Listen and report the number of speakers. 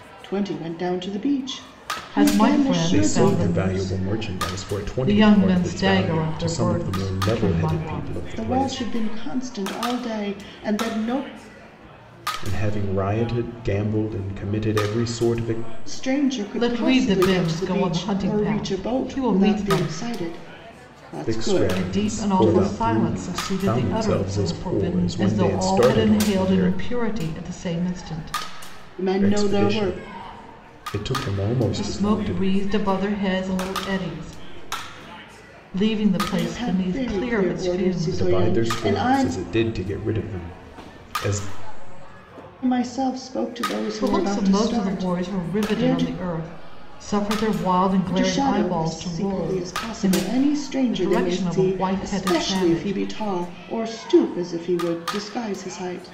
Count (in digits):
3